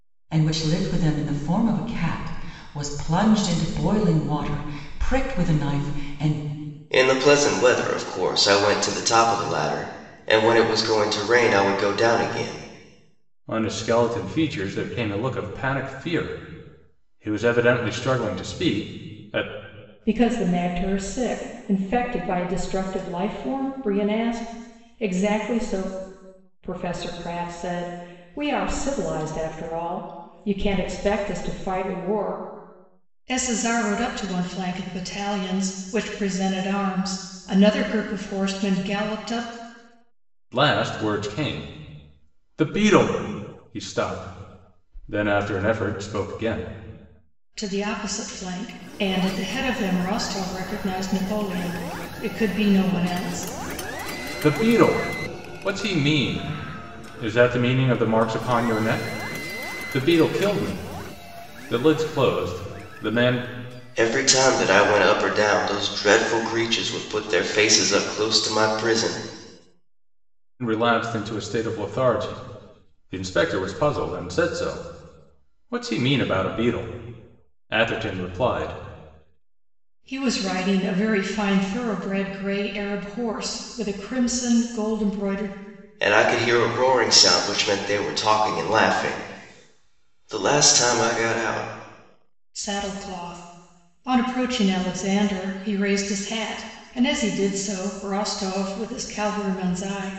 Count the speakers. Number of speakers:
four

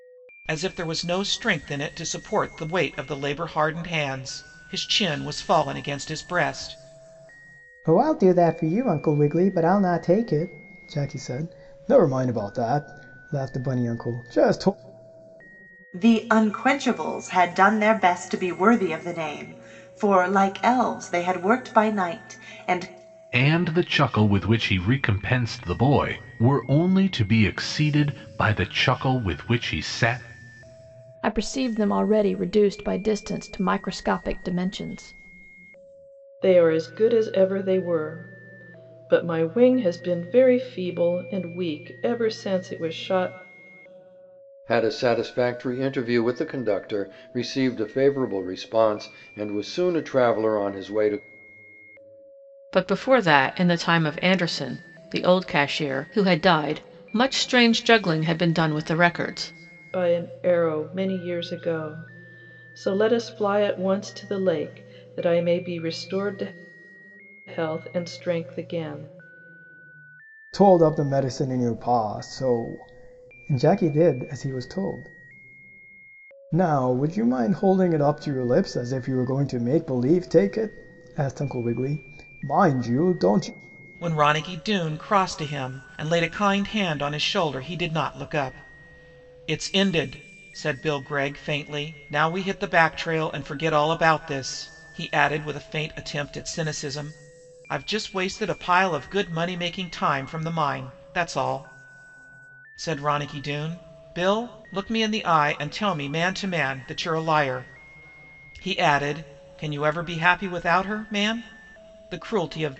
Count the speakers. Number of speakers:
eight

